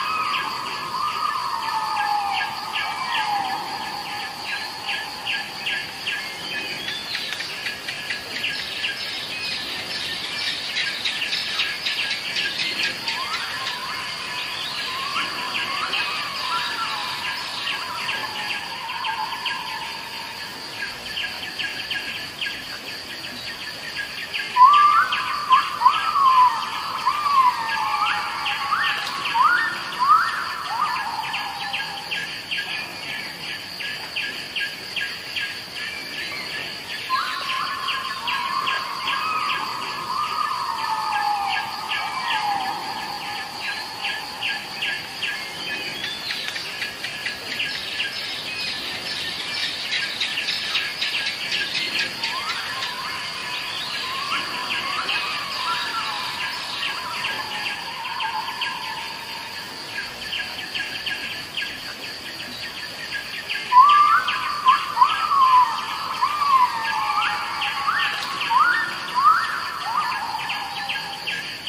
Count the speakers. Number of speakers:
zero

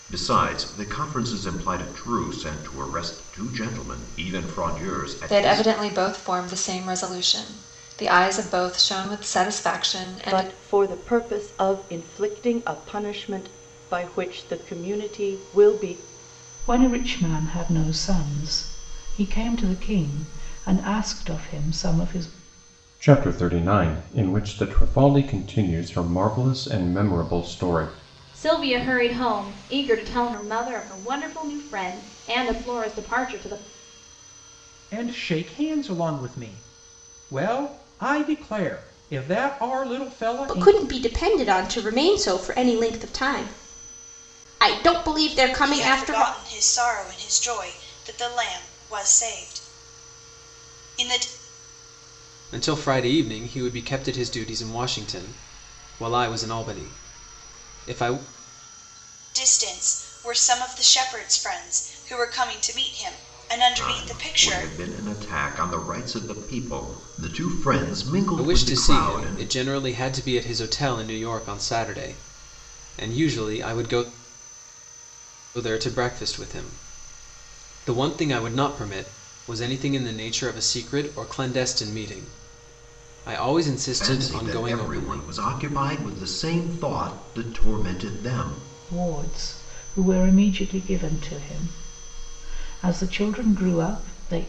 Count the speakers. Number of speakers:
ten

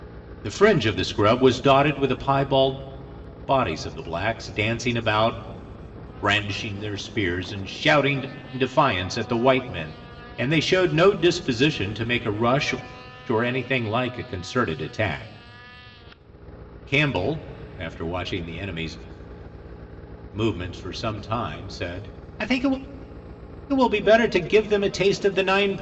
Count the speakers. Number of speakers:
one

